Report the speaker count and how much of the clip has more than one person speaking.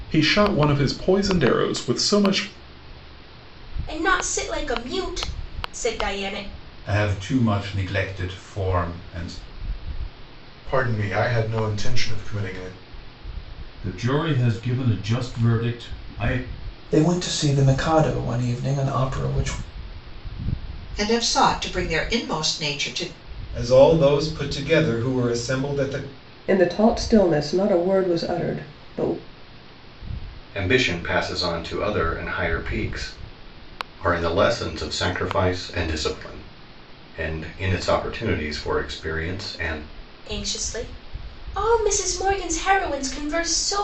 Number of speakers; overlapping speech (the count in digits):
10, no overlap